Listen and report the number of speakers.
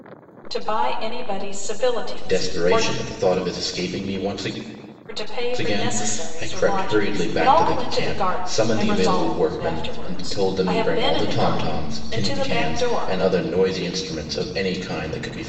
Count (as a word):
two